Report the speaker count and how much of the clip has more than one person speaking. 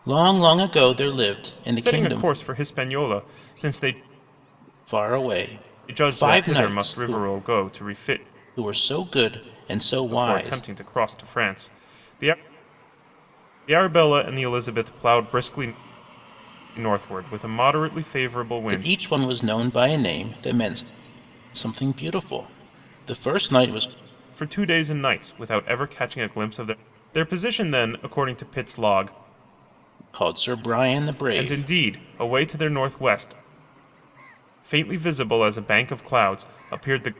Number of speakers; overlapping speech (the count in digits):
2, about 9%